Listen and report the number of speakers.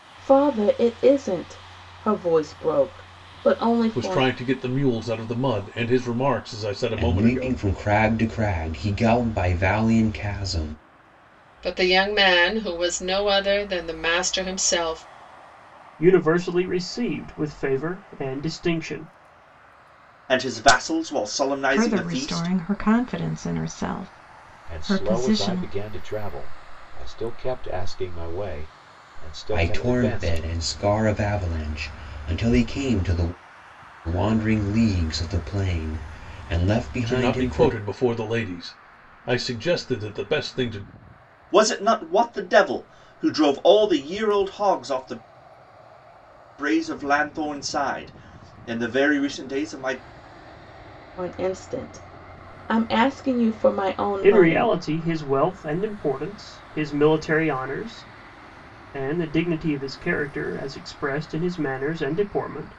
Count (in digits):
8